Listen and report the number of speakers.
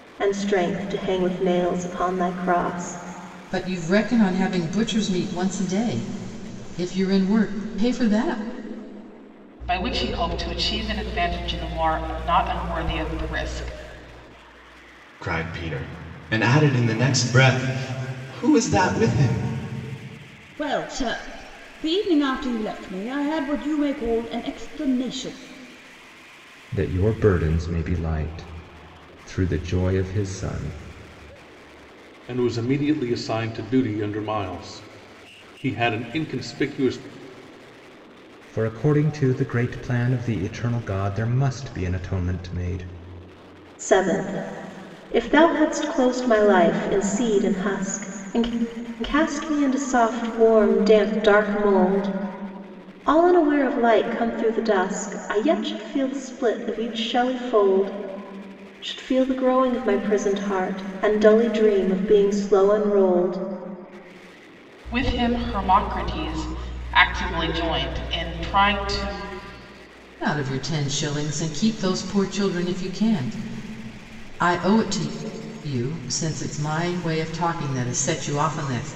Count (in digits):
7